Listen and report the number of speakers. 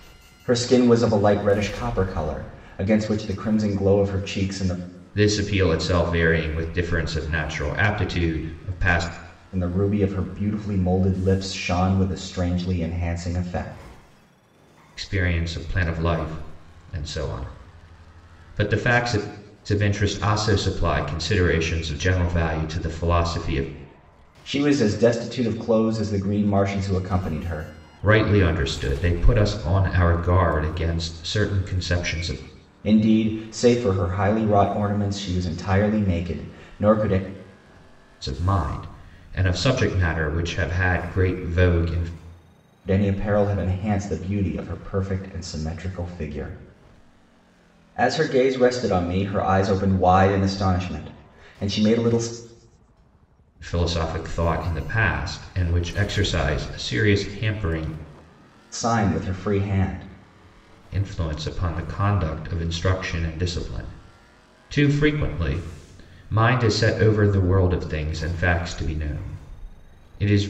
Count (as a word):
two